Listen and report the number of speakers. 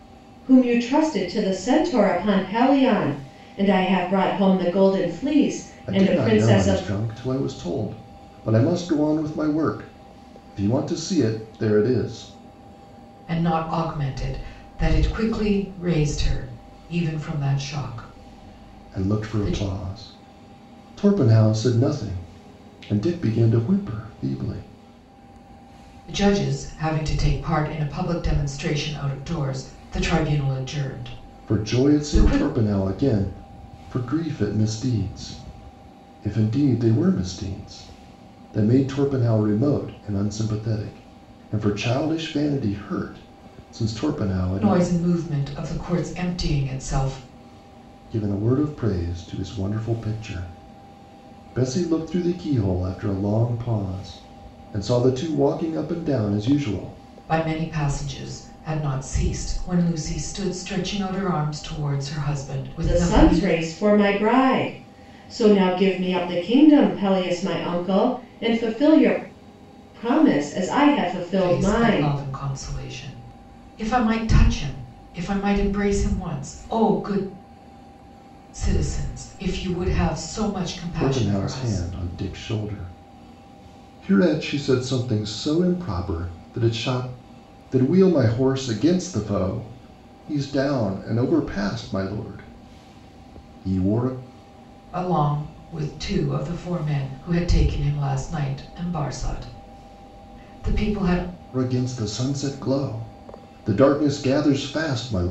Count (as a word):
three